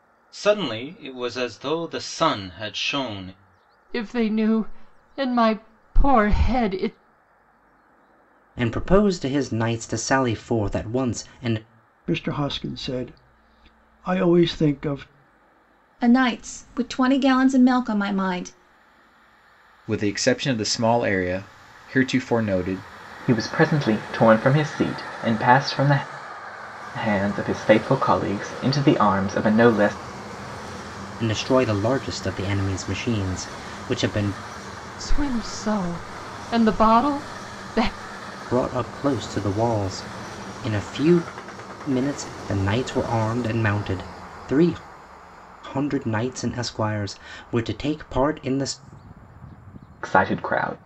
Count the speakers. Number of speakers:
7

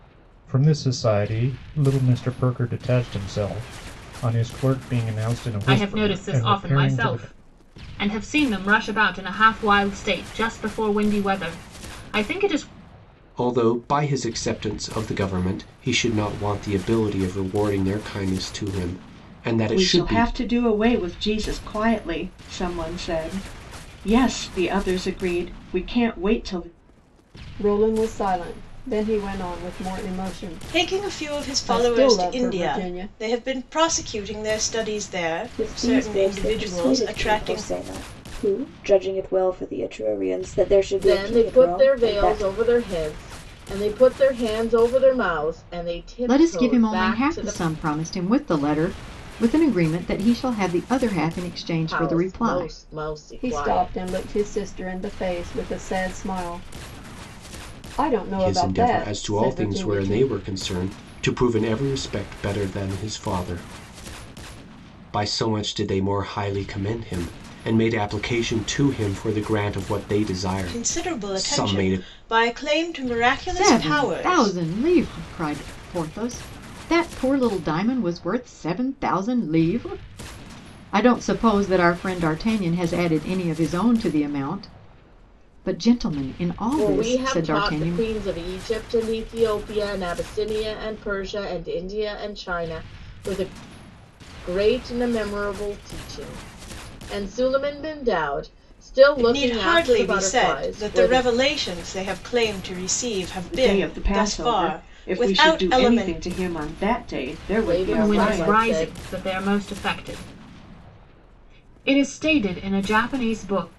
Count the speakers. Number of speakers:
9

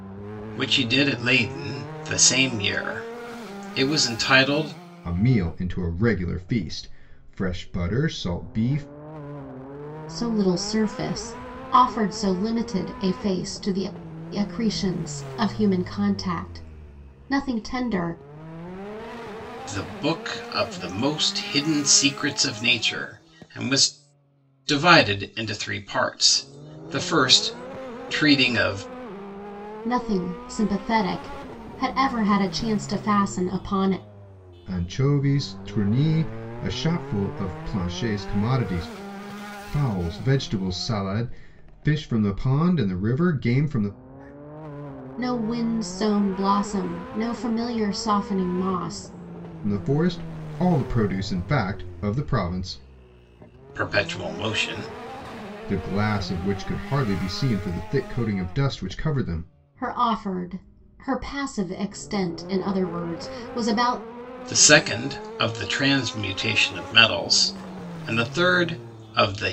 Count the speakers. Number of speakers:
3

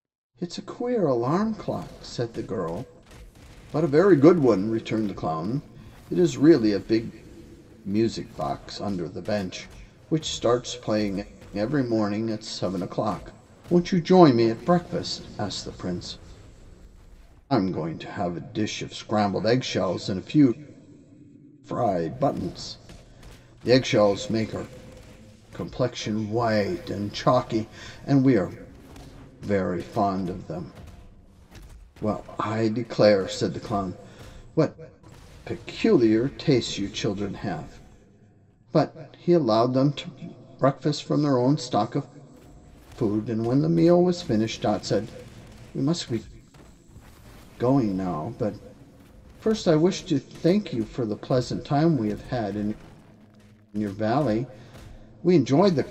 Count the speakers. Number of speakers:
1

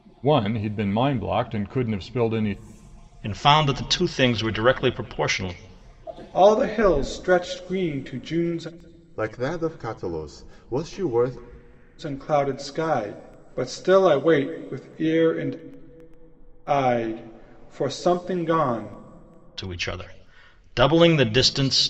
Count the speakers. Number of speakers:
4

